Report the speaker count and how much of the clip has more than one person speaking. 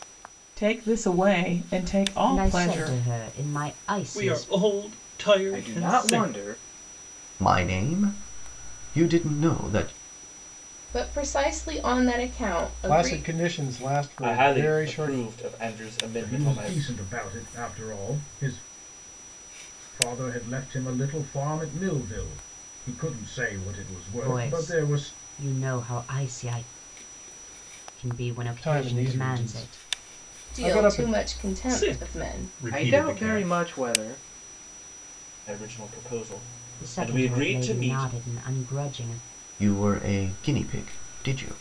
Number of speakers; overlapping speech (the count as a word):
nine, about 25%